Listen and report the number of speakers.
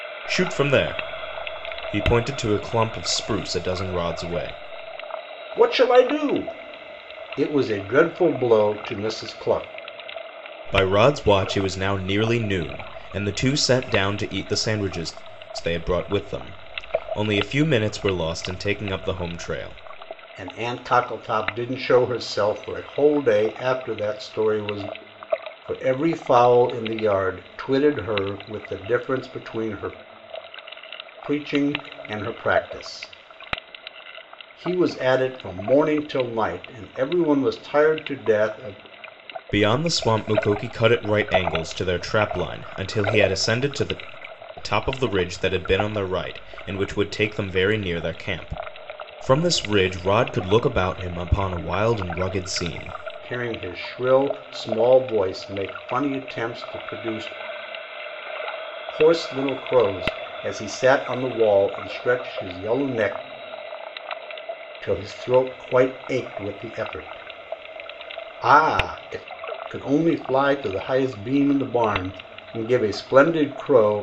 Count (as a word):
two